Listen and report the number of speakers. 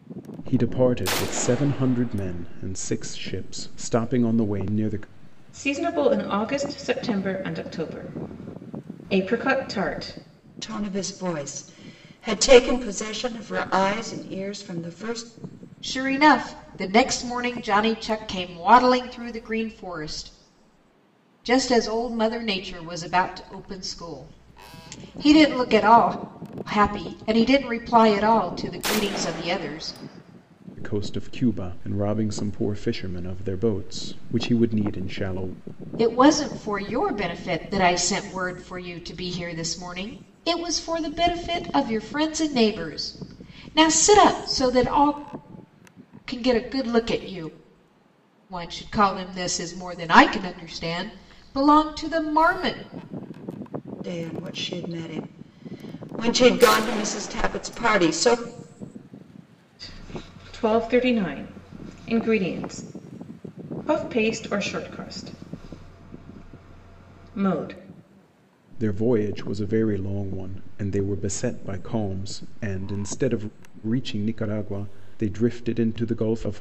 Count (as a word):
four